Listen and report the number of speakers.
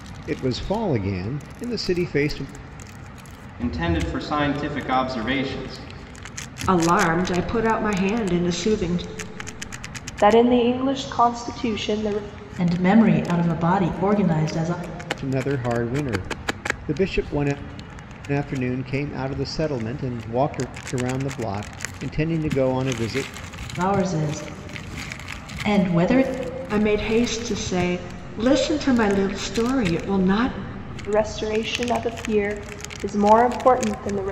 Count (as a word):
five